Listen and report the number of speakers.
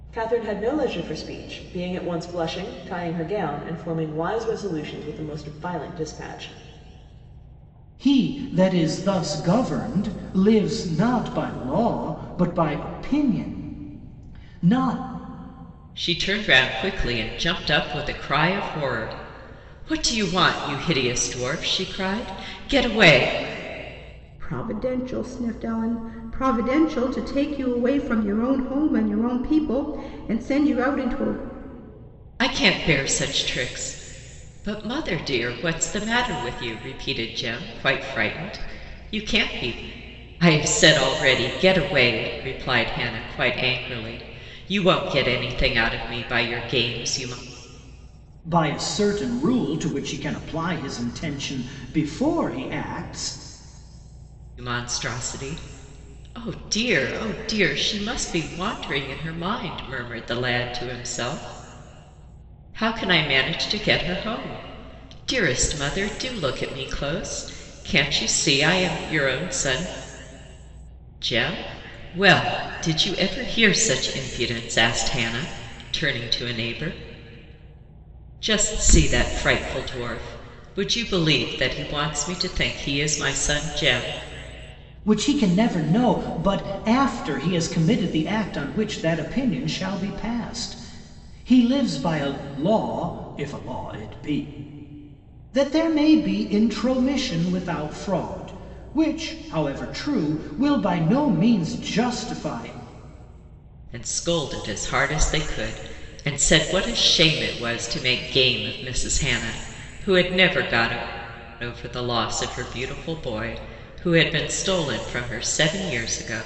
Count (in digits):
4